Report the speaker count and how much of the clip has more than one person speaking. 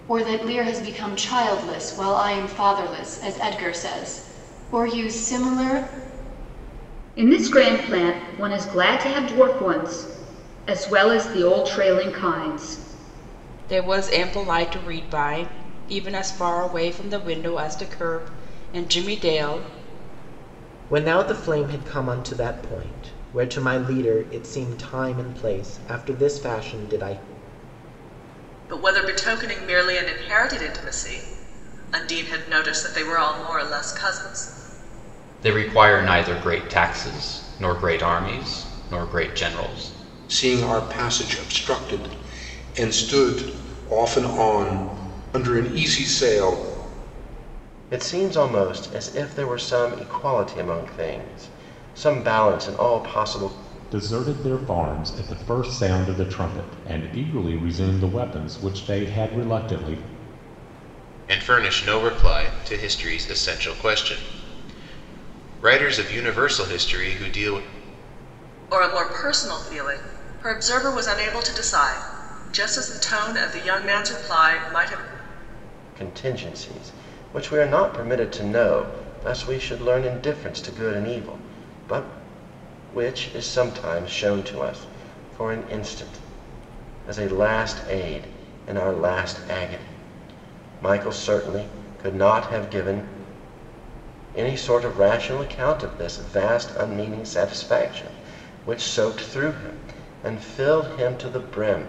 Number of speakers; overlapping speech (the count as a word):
ten, no overlap